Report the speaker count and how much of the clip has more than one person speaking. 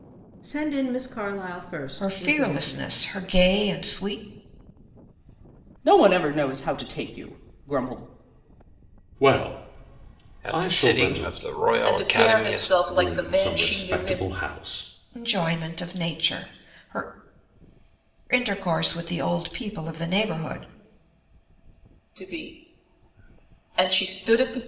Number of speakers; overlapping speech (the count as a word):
six, about 17%